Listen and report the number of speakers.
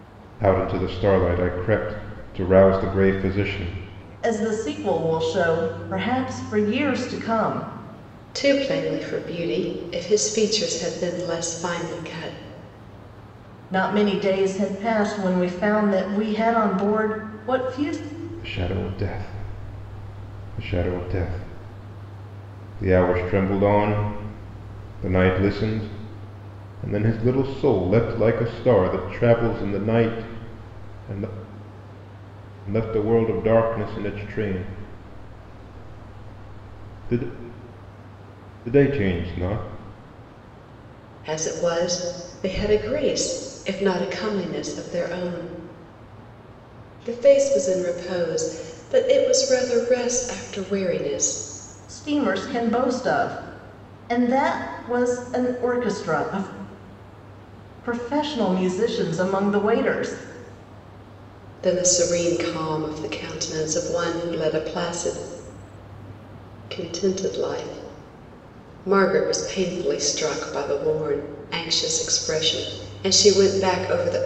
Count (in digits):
3